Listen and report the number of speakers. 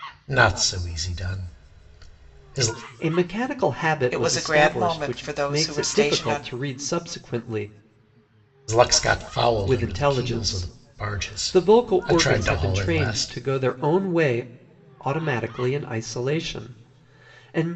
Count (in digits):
3